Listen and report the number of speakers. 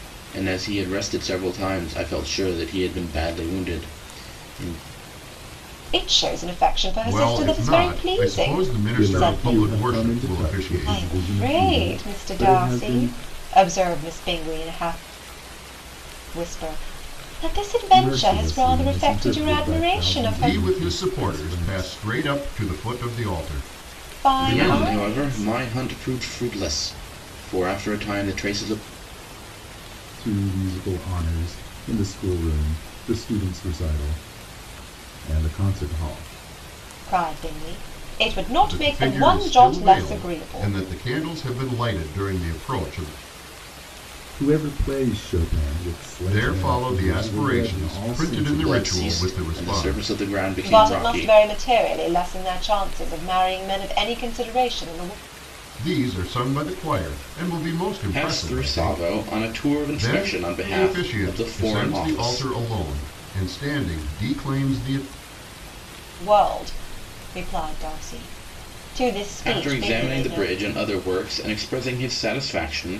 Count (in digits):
4